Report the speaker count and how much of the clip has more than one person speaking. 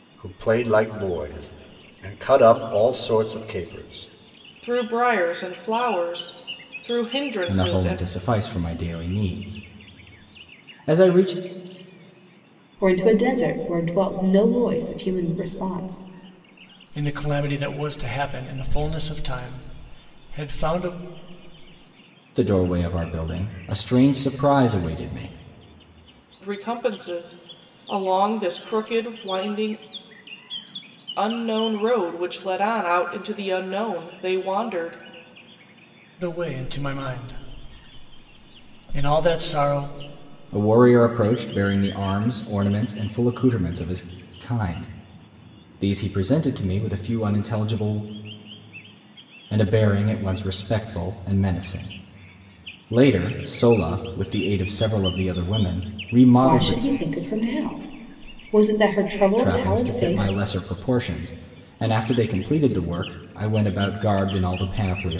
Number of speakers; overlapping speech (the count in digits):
5, about 3%